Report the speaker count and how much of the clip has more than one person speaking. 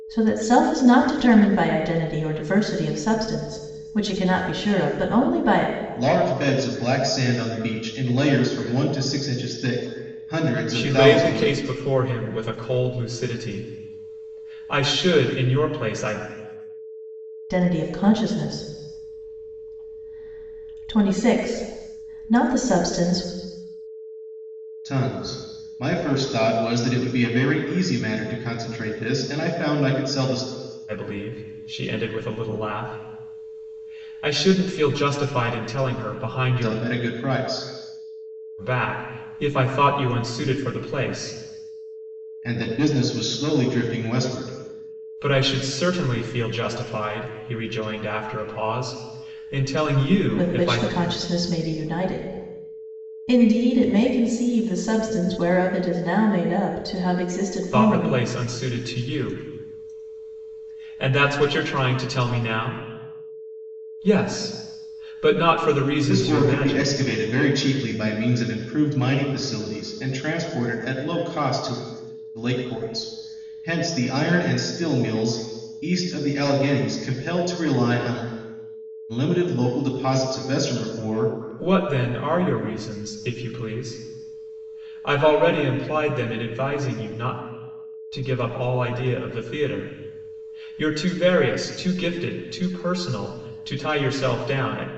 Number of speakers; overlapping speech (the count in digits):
3, about 4%